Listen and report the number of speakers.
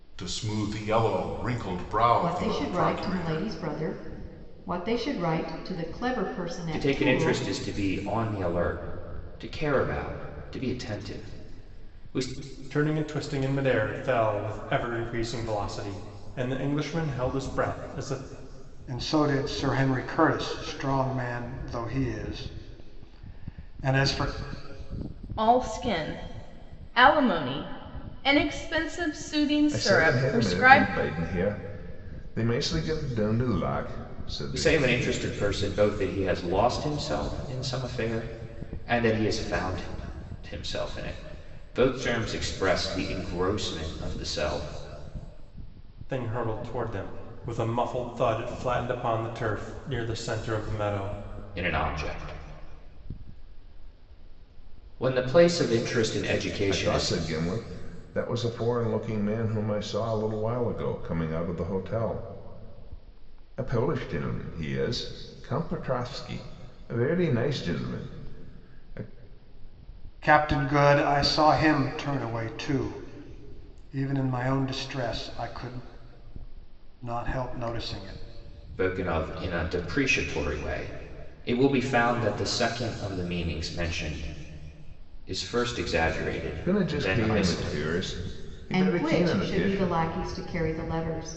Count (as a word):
seven